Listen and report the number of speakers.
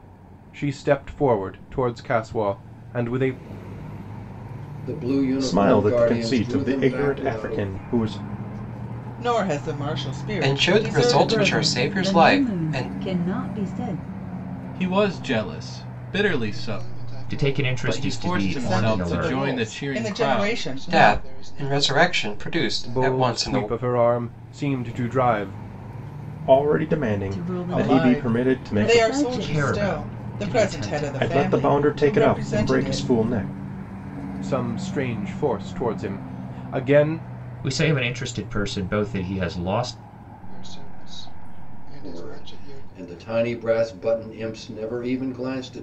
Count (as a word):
nine